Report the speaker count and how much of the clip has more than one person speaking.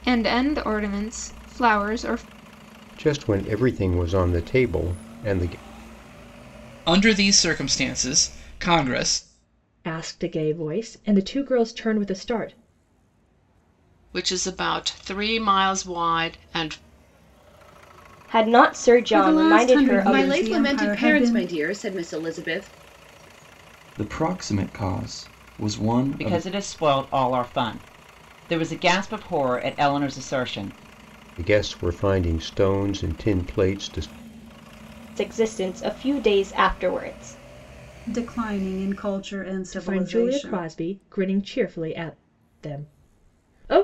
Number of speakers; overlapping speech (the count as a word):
ten, about 9%